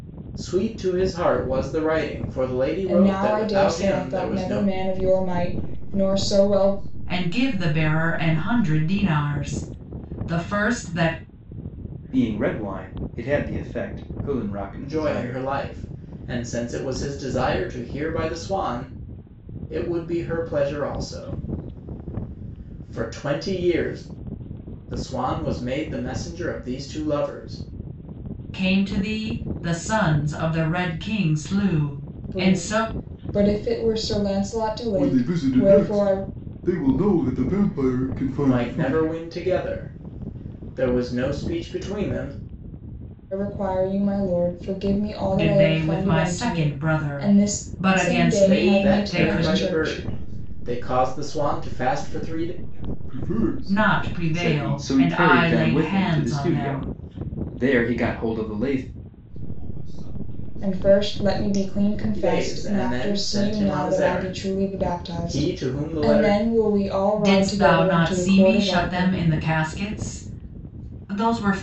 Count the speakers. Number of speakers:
five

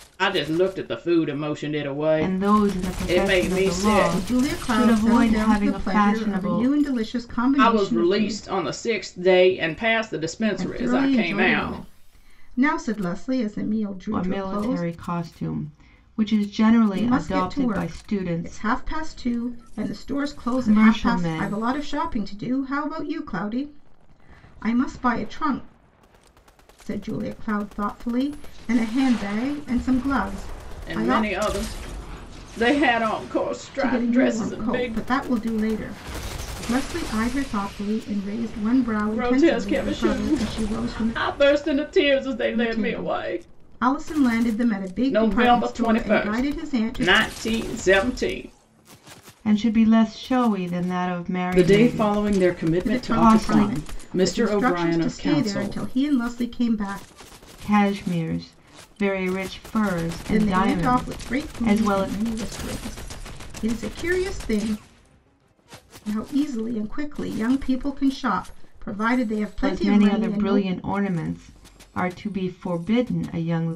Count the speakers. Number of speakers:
three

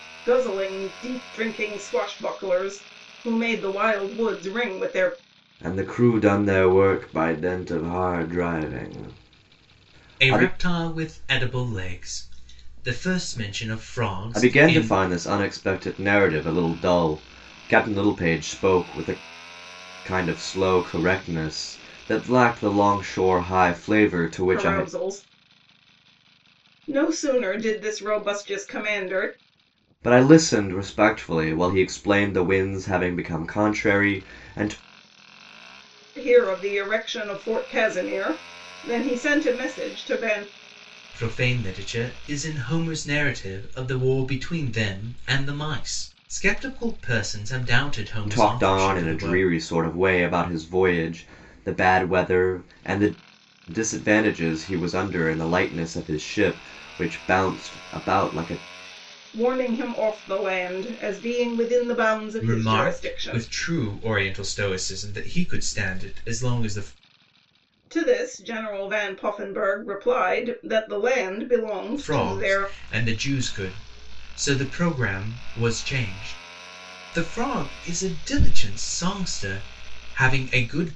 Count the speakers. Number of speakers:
three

